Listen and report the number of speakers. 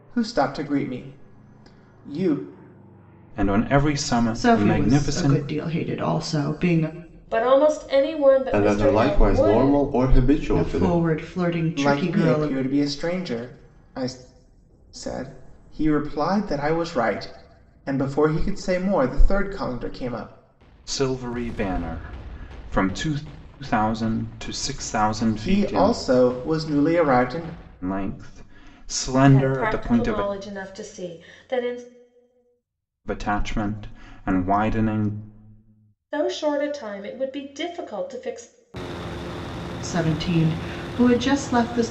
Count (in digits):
5